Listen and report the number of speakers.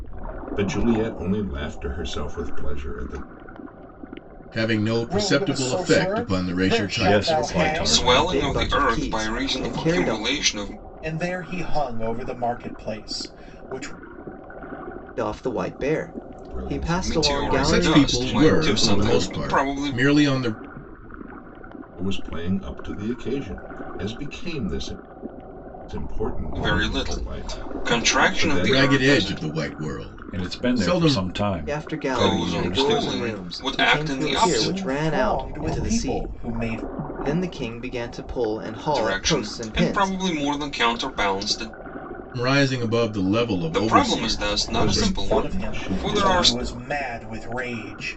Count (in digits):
6